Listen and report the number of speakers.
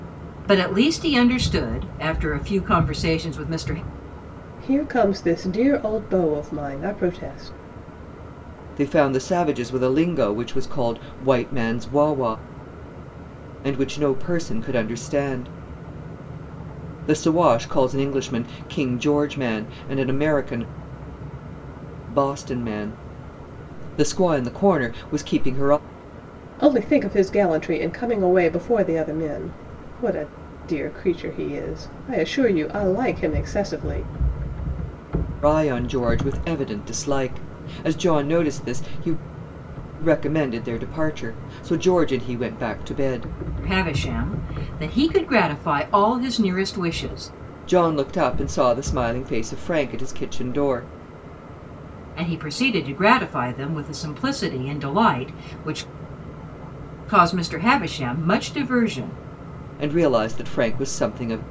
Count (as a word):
three